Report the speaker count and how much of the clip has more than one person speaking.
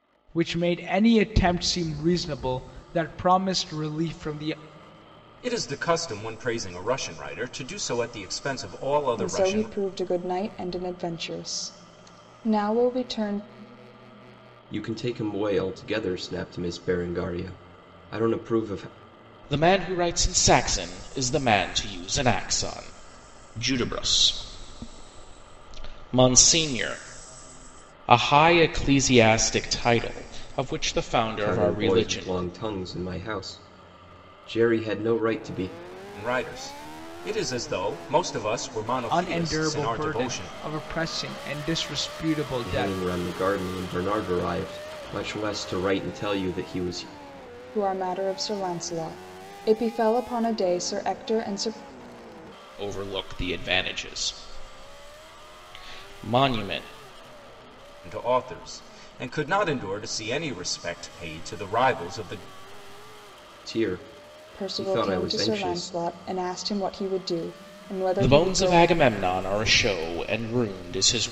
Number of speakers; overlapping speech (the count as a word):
five, about 8%